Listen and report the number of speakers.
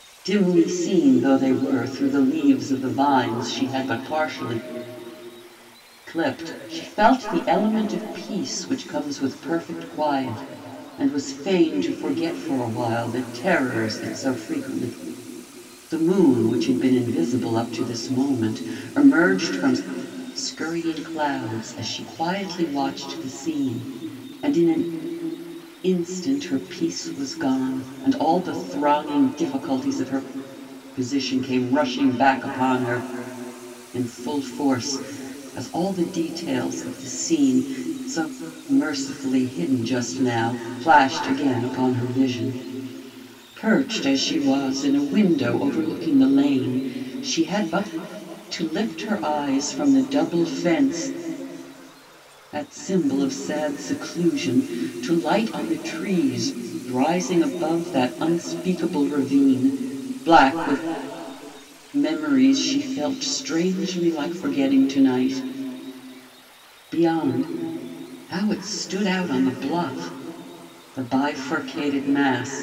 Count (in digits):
1